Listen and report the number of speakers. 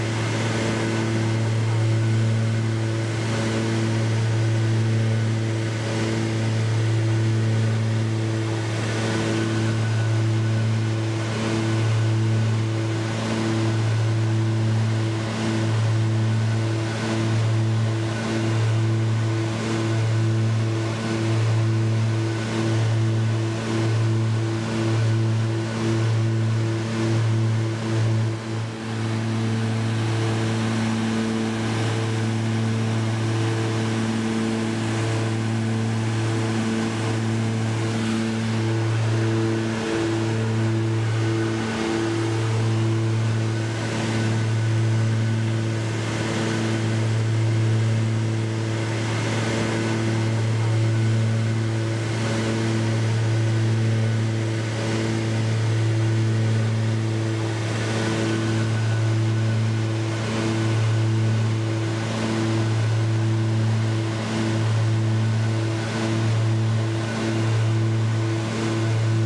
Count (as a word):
zero